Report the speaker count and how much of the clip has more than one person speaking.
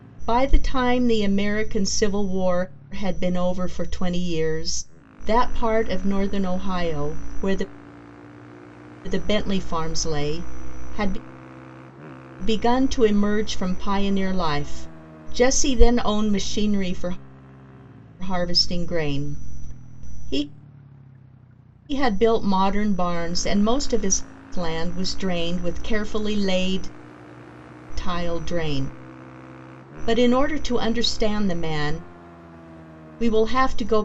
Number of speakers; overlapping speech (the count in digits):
1, no overlap